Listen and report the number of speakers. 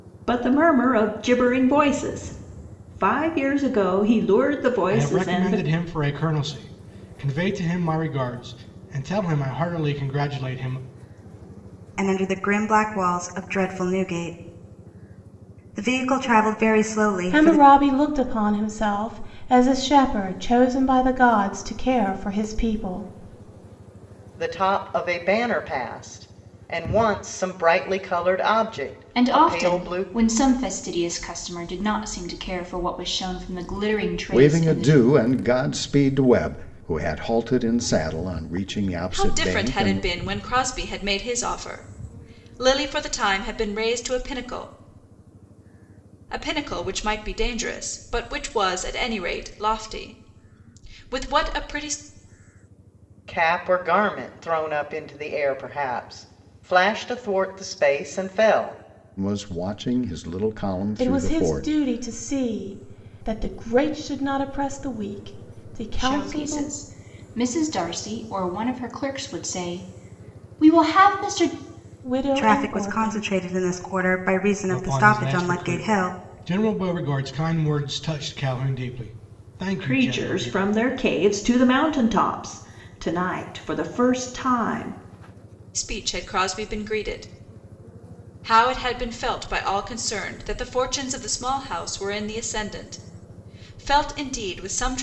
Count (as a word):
eight